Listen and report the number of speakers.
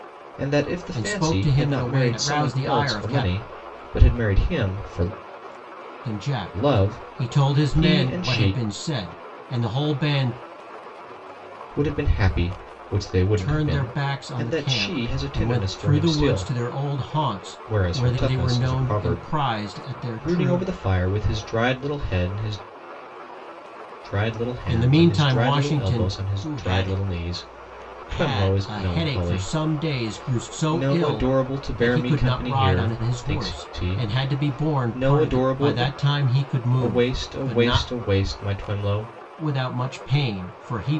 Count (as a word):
two